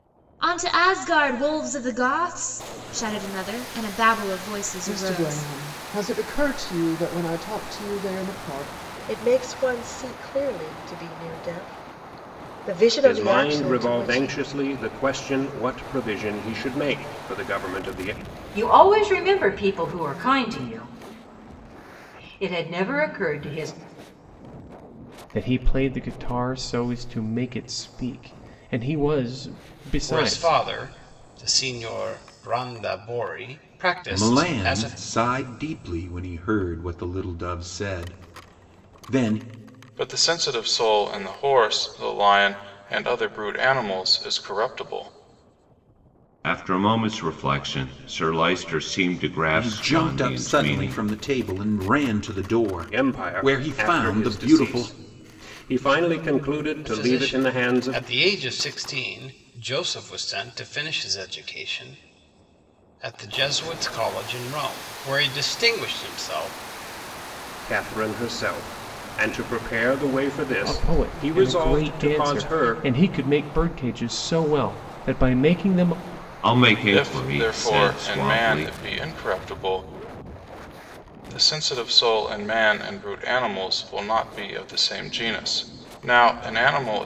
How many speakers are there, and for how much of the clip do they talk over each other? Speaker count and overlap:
ten, about 14%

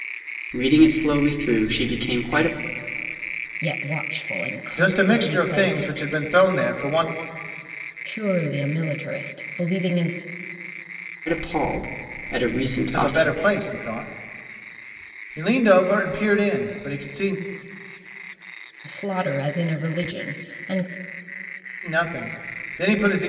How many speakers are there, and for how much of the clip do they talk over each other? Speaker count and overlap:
three, about 7%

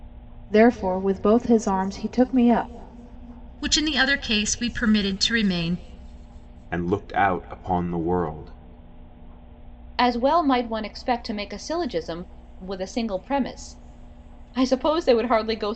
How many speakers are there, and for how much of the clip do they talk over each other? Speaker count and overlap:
four, no overlap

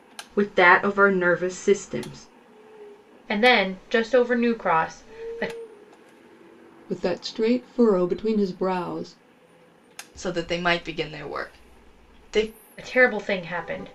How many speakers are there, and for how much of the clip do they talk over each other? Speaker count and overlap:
four, no overlap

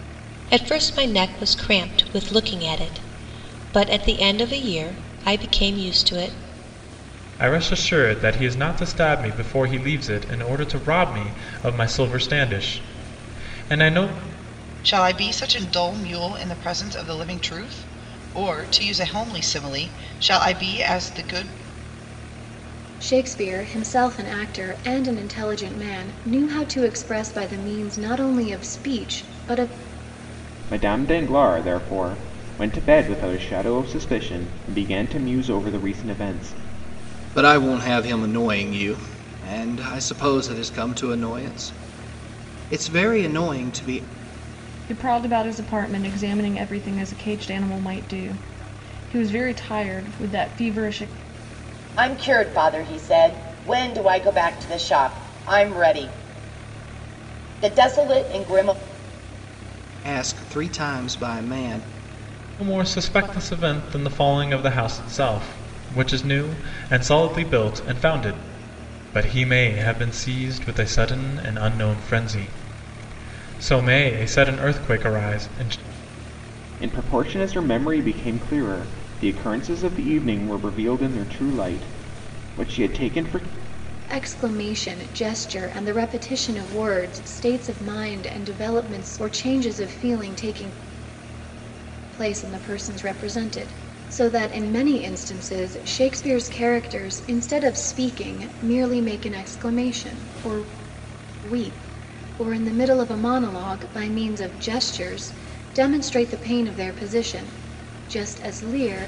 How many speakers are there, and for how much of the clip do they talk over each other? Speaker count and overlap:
eight, no overlap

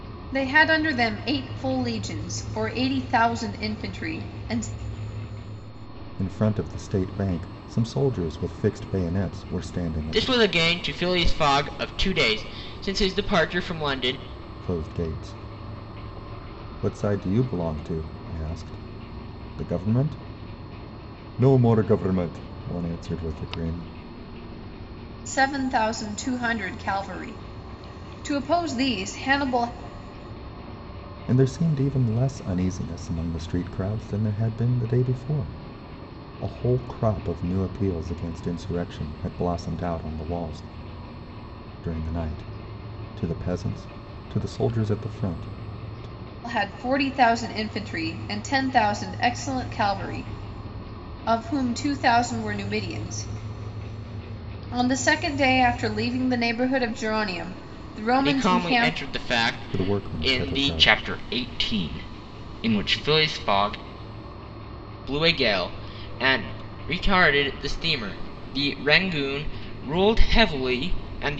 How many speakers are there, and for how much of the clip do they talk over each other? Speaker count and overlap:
three, about 4%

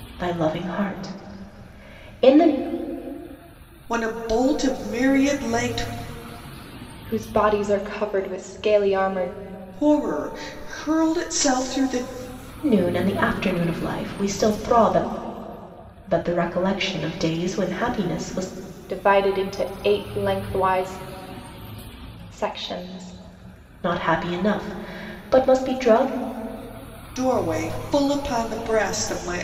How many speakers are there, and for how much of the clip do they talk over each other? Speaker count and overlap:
three, no overlap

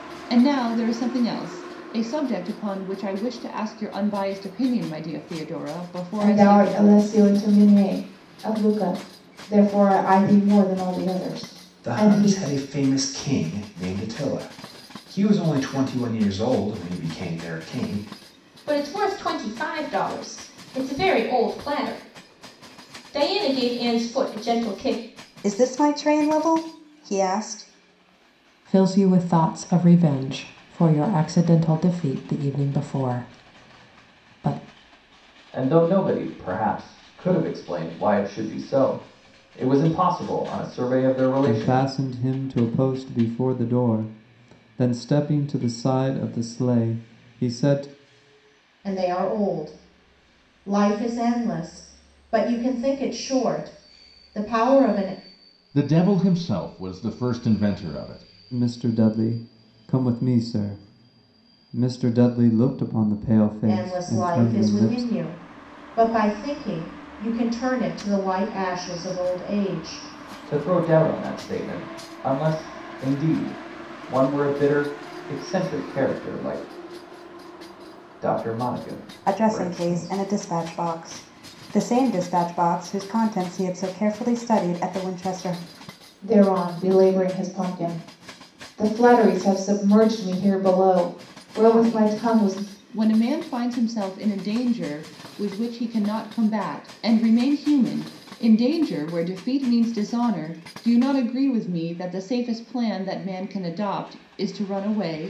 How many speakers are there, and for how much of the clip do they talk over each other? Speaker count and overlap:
ten, about 5%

